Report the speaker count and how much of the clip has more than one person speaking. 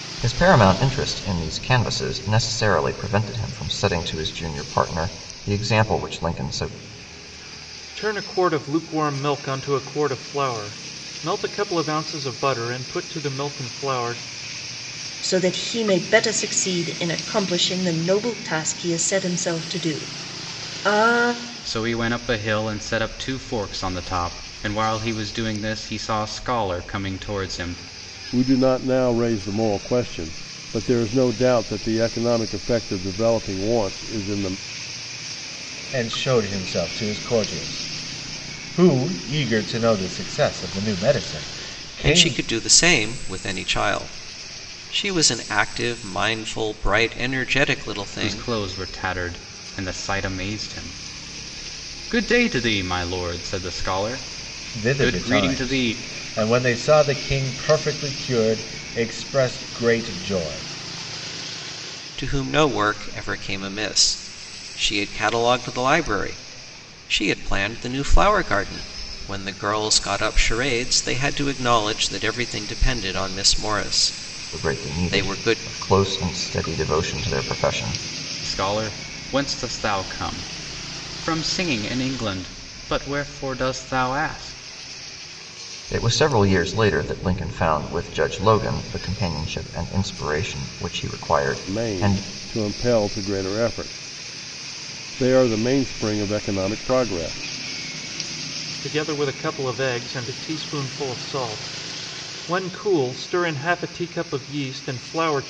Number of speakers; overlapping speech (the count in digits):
7, about 3%